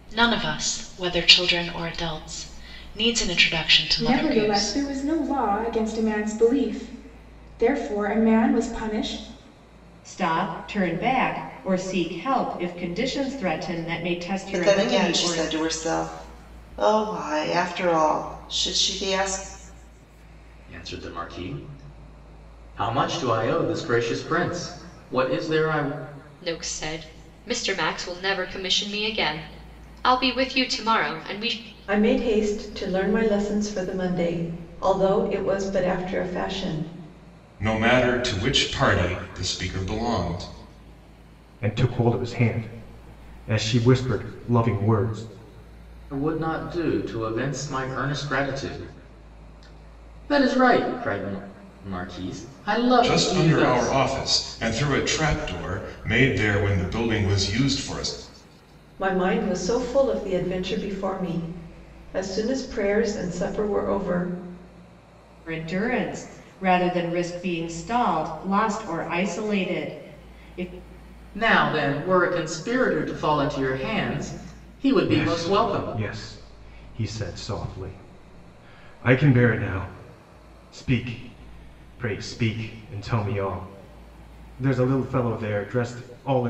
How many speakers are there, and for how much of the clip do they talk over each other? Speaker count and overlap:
9, about 4%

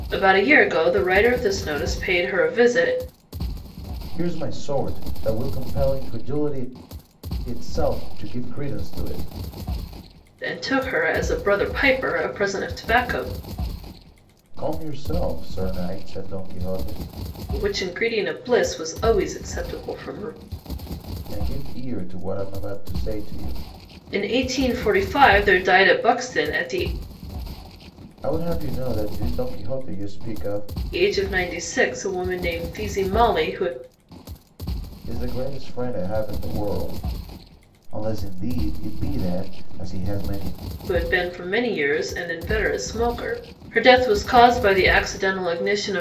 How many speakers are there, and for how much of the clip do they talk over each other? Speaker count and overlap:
2, no overlap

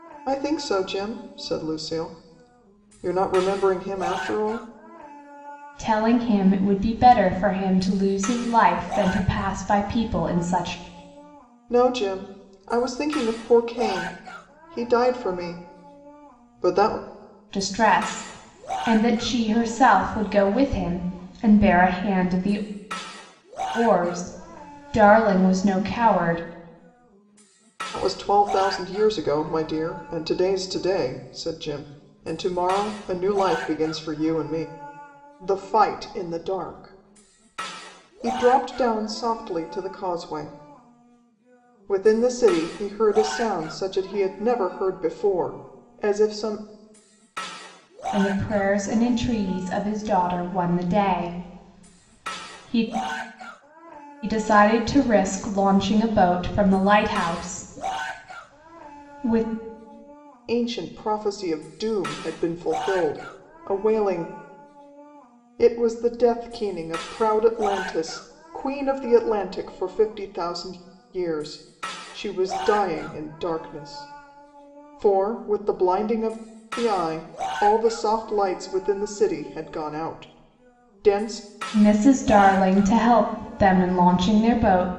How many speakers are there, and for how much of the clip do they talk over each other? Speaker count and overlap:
2, no overlap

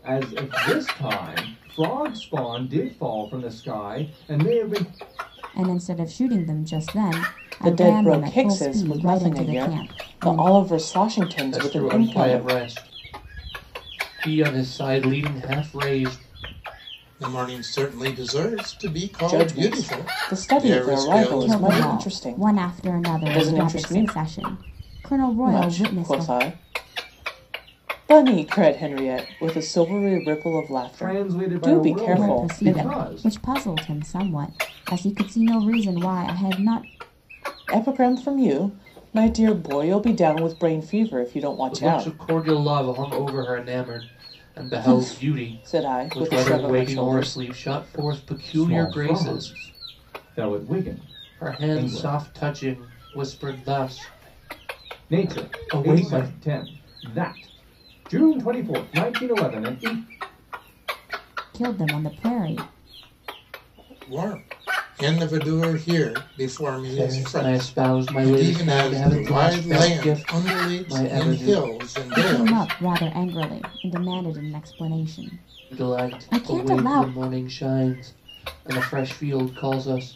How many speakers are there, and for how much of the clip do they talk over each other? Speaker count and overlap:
5, about 32%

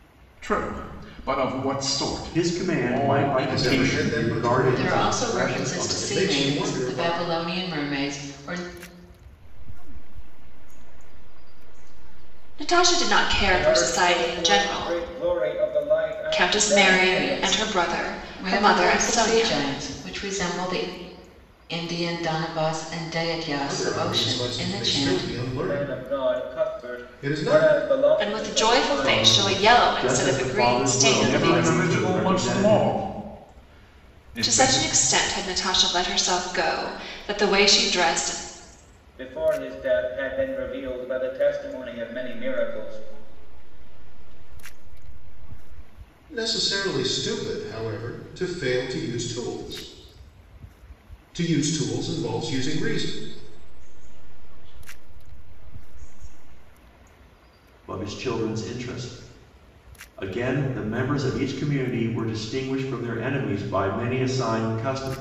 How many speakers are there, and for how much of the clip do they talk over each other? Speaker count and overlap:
7, about 33%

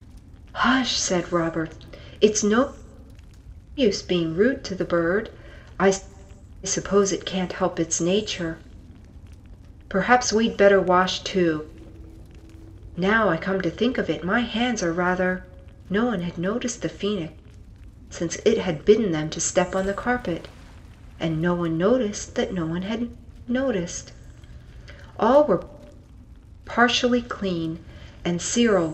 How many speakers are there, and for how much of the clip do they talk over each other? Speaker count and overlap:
1, no overlap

